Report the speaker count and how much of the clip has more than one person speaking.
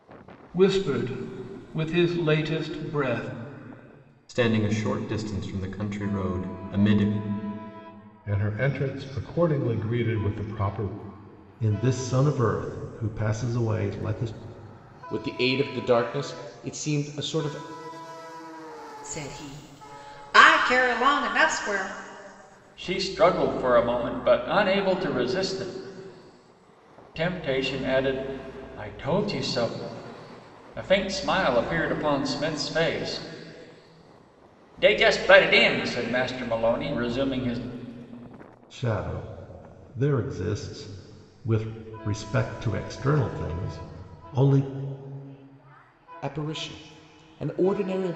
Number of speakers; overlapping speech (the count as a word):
seven, no overlap